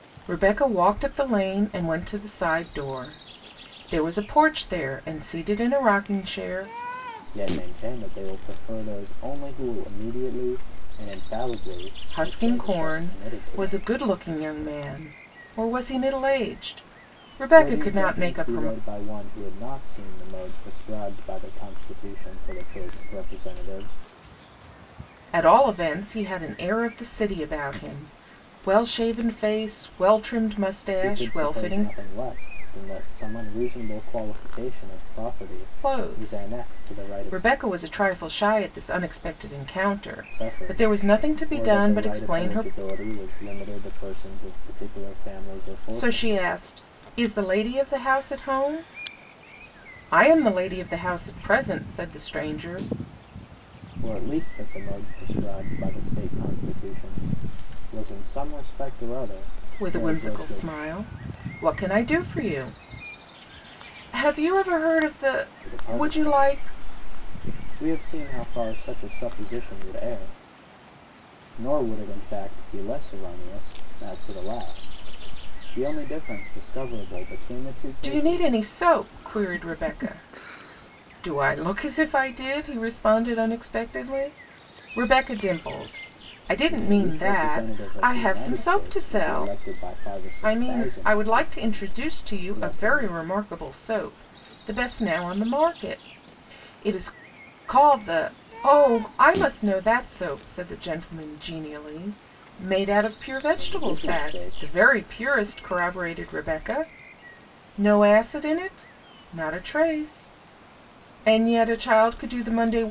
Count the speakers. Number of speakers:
two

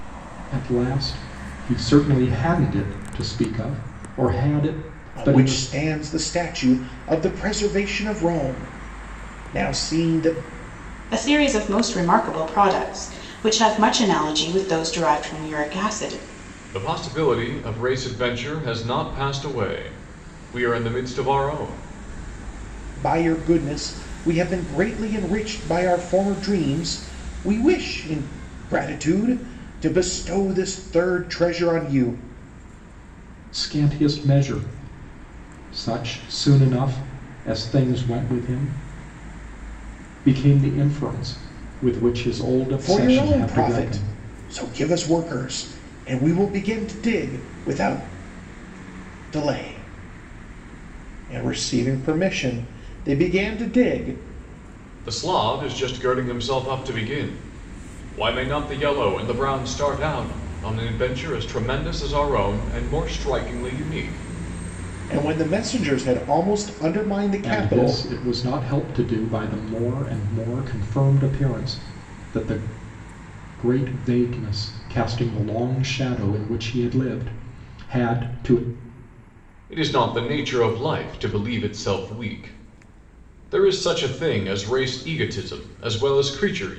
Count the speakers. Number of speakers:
four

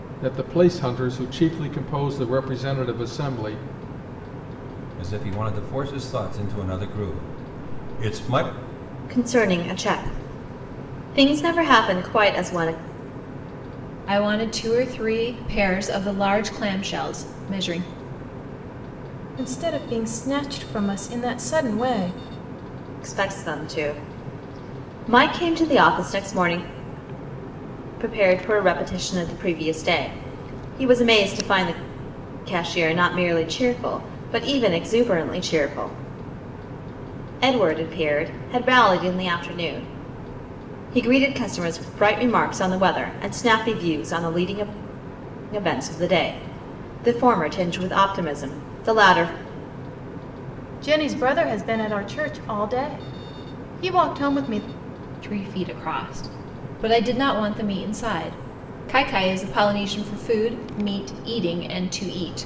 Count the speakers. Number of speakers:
five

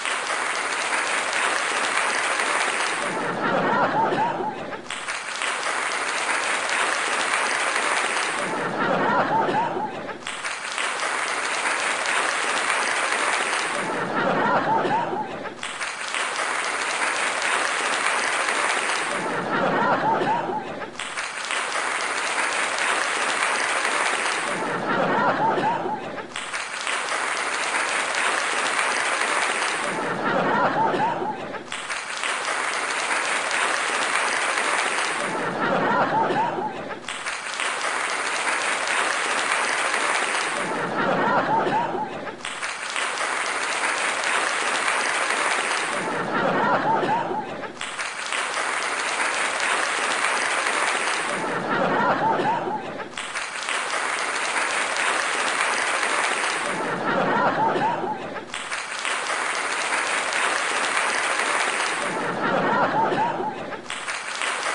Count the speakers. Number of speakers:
zero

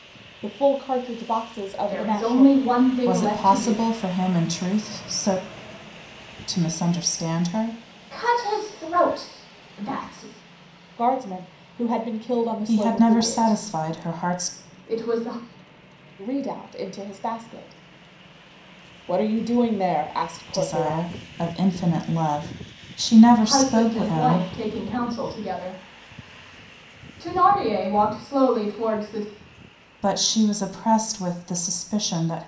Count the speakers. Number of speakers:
three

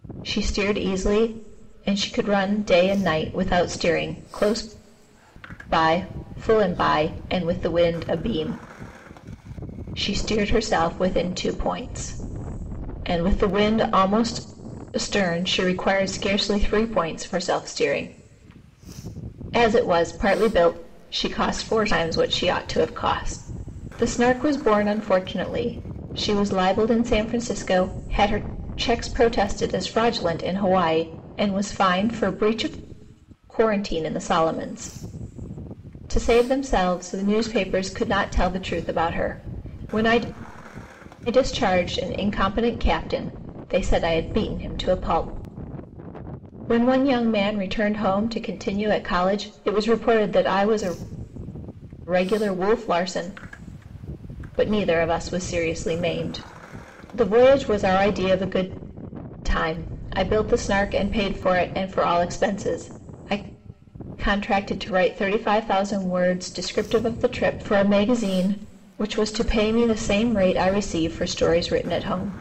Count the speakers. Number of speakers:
one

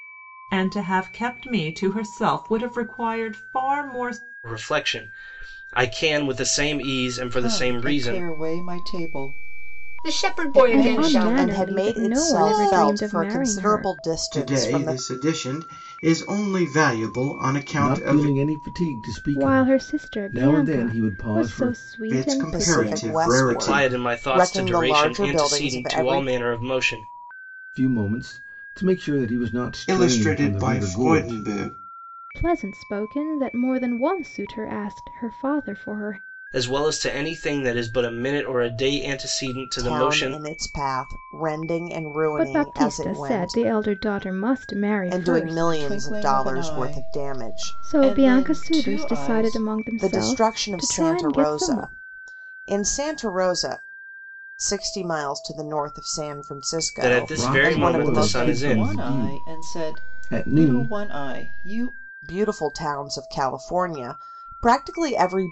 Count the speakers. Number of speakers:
eight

